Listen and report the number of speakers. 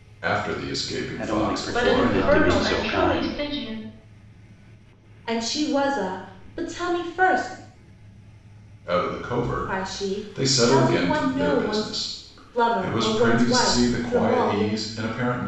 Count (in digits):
4